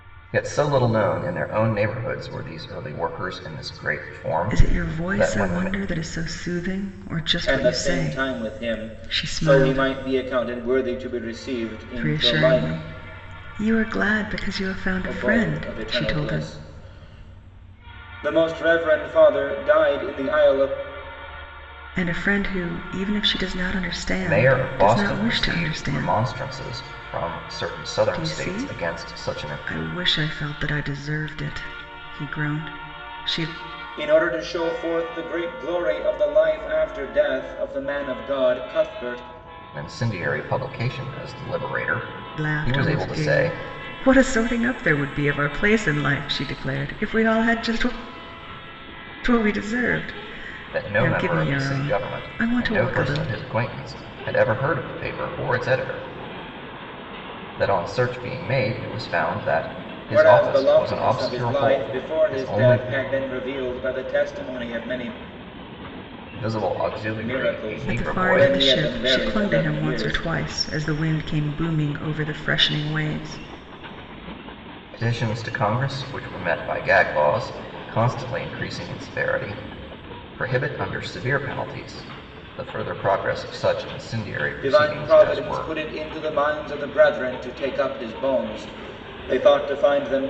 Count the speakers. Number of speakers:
3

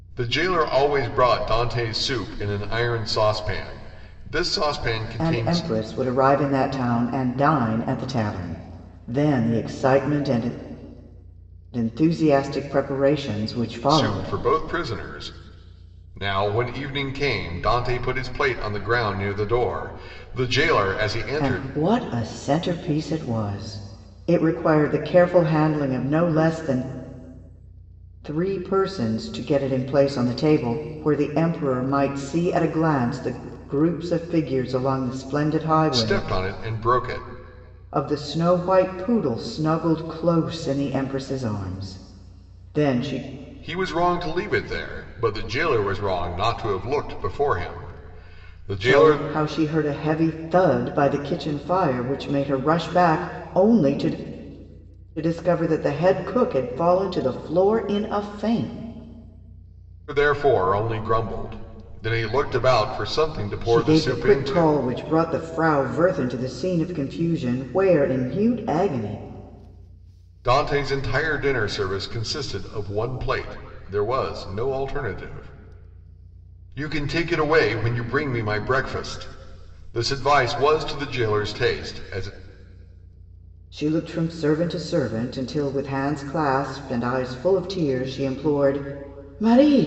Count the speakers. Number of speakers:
2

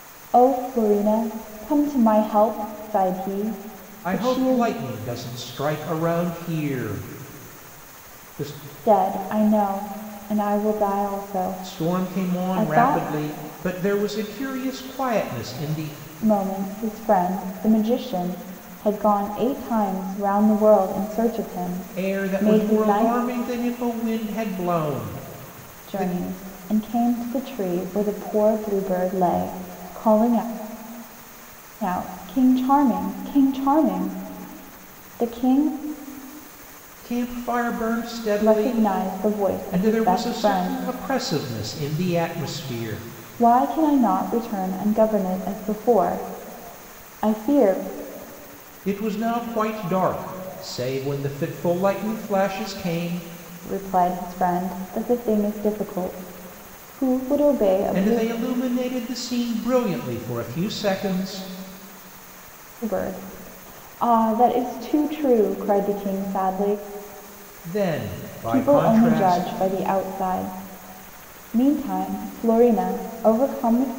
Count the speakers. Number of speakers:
2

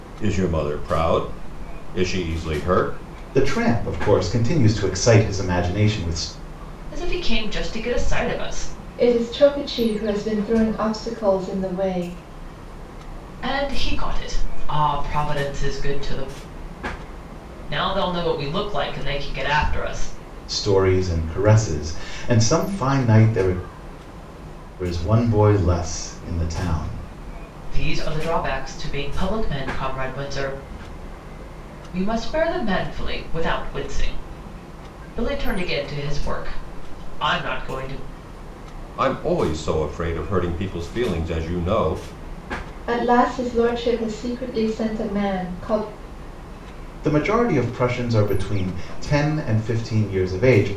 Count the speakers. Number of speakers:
4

